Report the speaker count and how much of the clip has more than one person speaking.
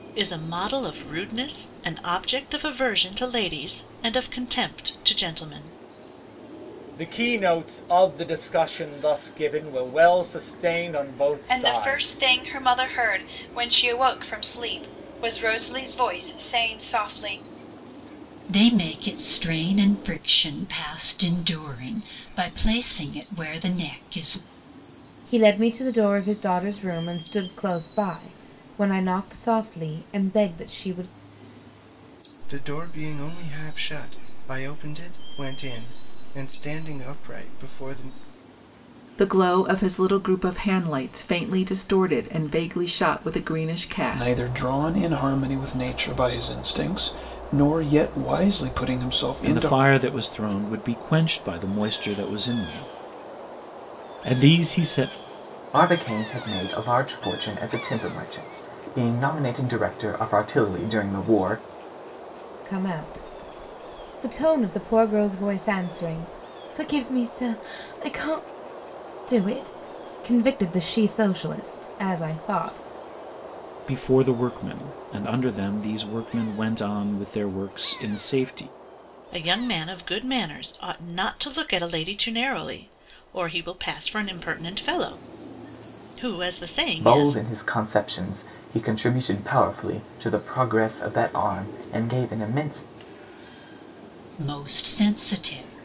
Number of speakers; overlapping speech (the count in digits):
10, about 2%